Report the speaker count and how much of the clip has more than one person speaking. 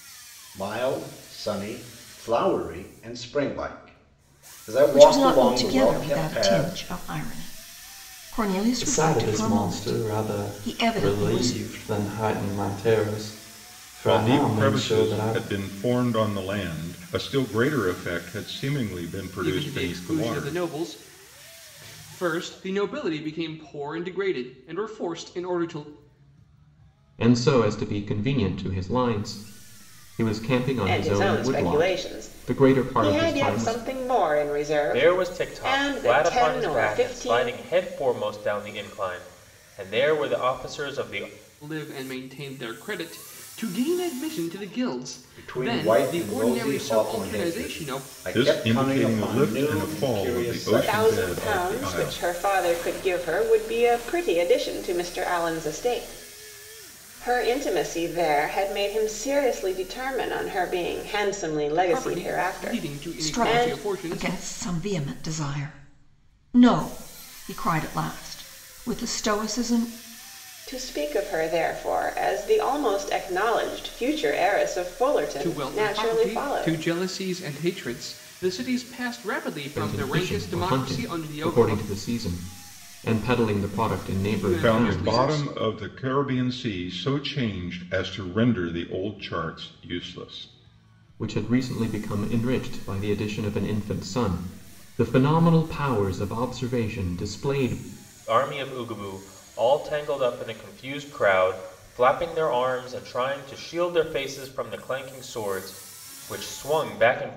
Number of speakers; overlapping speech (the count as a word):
eight, about 26%